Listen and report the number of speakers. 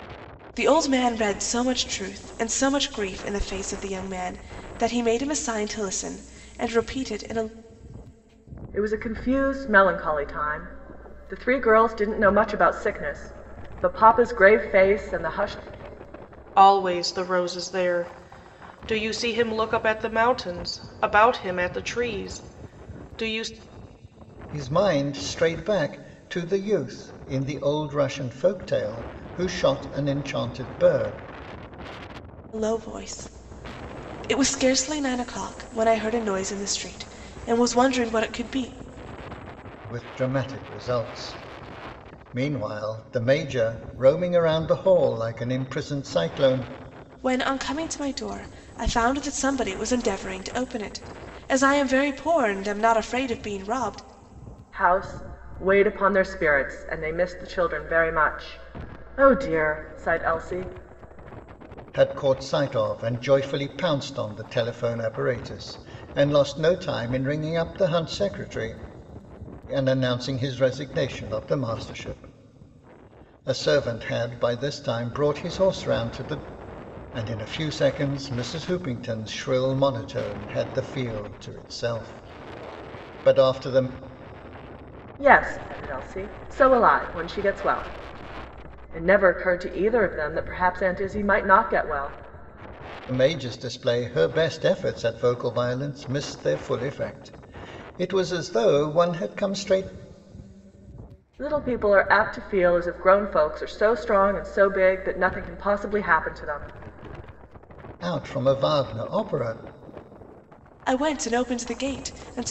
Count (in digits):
4